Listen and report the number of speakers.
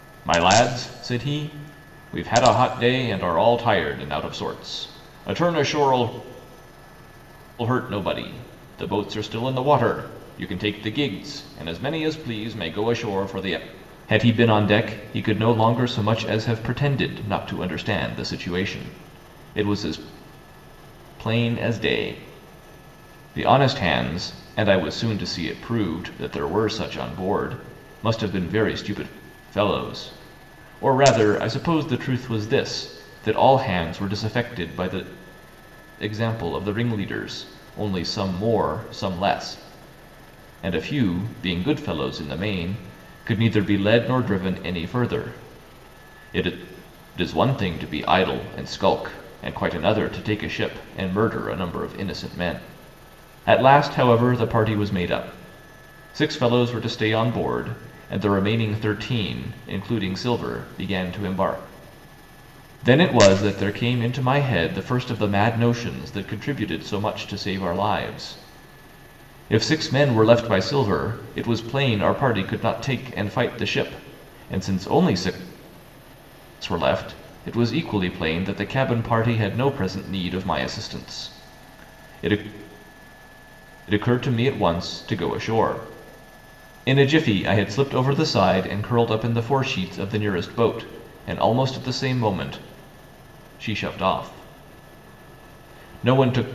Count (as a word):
one